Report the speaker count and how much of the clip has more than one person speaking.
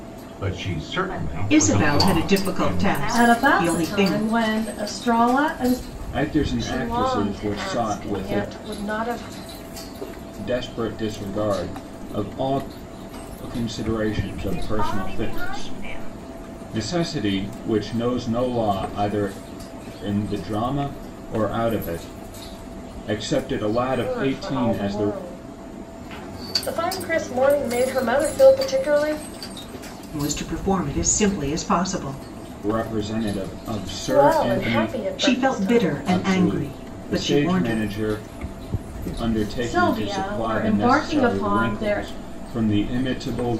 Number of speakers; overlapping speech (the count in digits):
6, about 32%